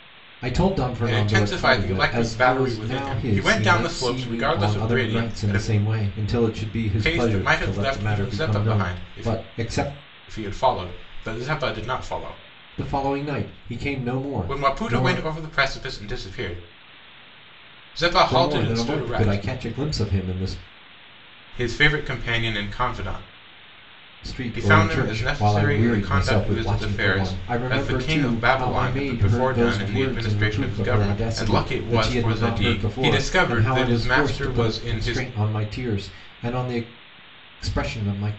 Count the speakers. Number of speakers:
2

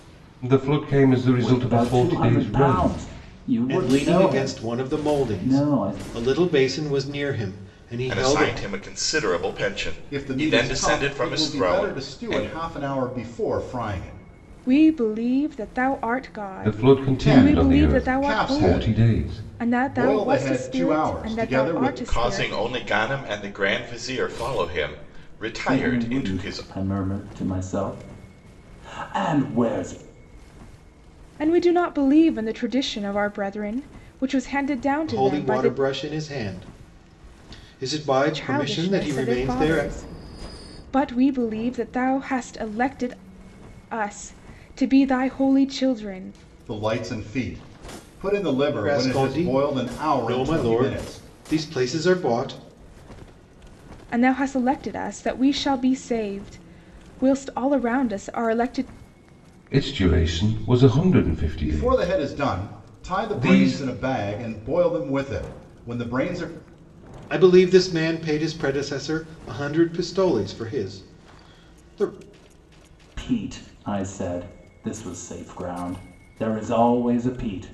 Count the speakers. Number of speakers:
6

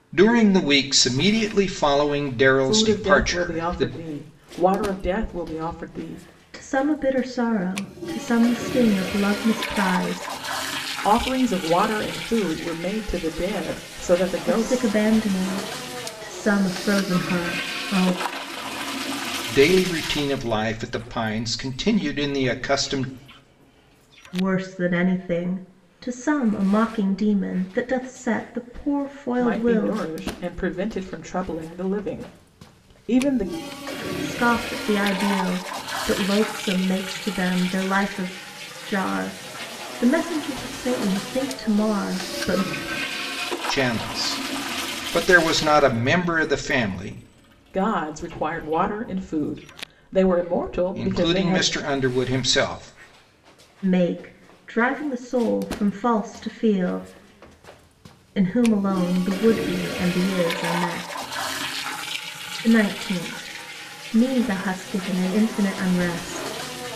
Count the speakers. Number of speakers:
3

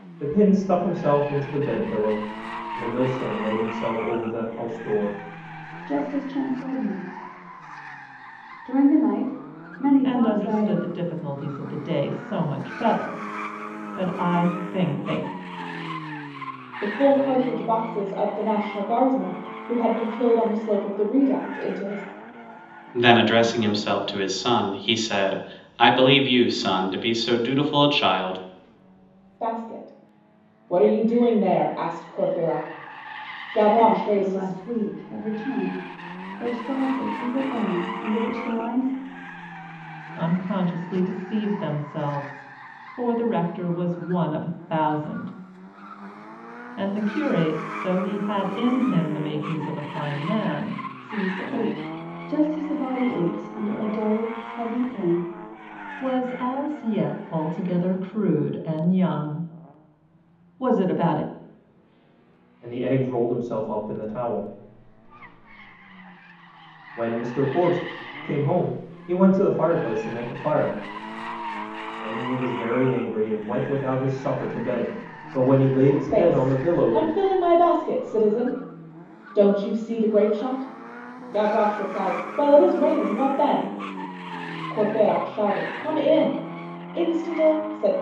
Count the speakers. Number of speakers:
5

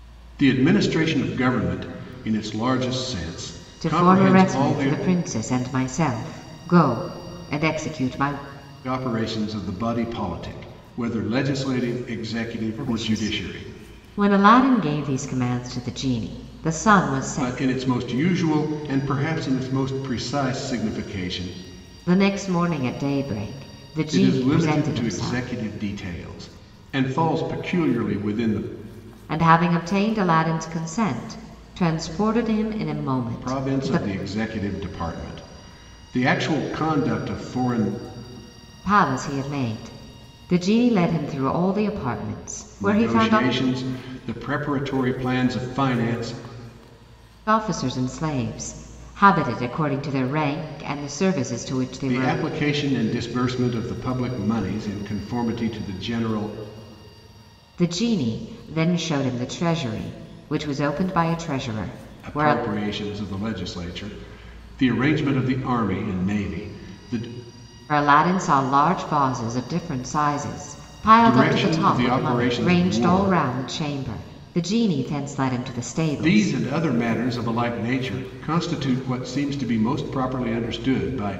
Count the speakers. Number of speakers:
2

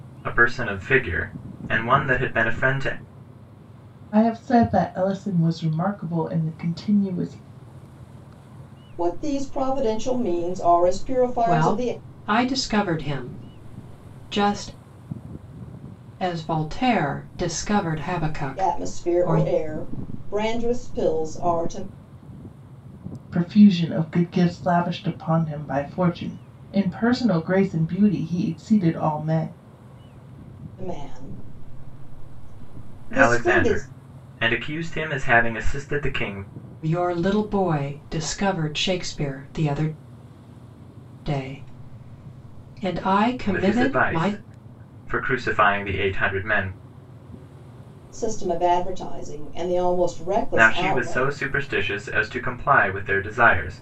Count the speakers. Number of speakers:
4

